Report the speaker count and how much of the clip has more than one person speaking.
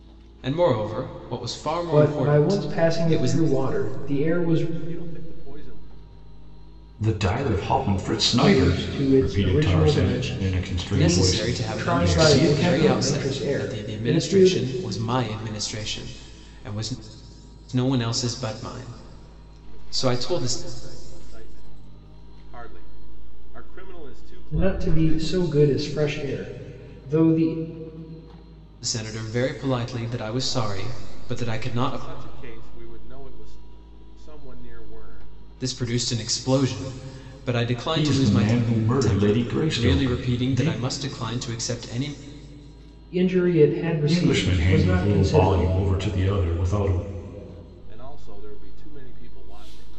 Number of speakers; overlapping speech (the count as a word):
four, about 33%